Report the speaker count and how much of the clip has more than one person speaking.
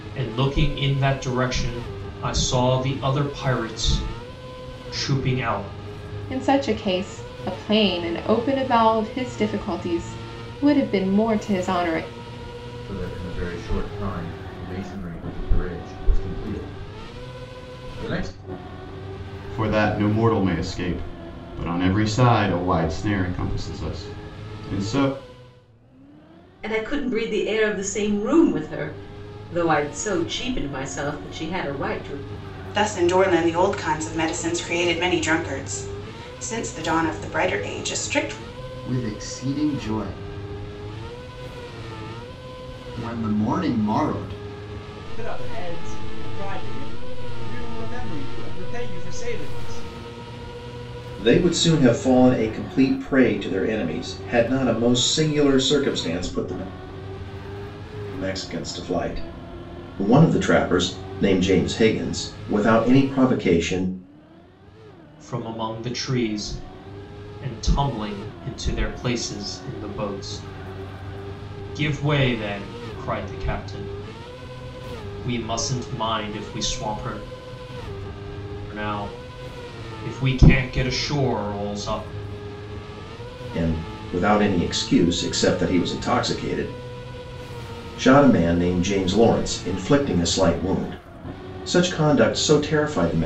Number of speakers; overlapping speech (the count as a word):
nine, no overlap